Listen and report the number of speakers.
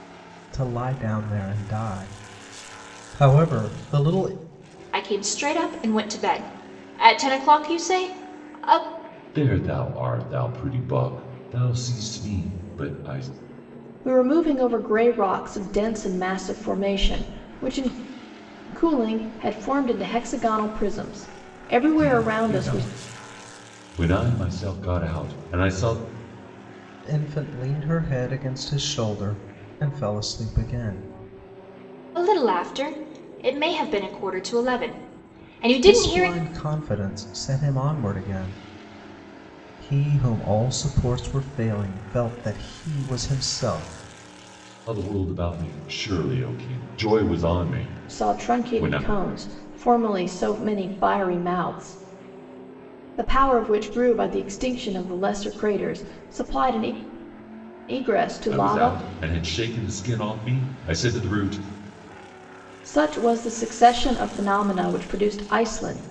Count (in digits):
4